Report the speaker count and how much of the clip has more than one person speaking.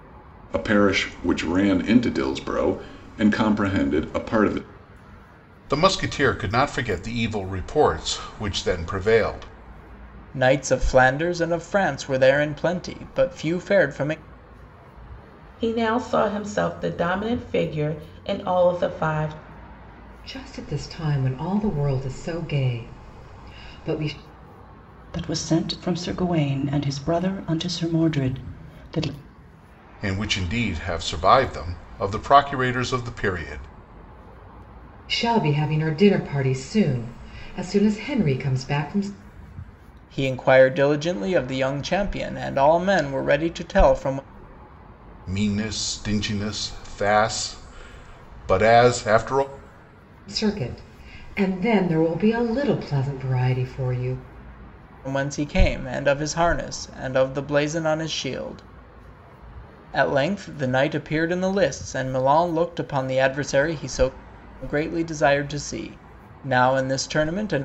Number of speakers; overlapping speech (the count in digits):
6, no overlap